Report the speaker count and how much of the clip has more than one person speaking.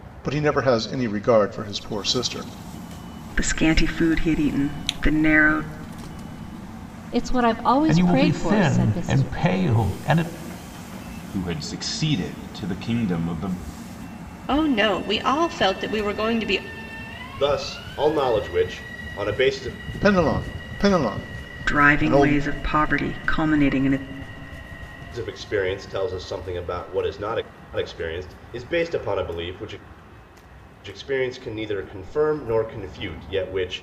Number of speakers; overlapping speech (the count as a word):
seven, about 7%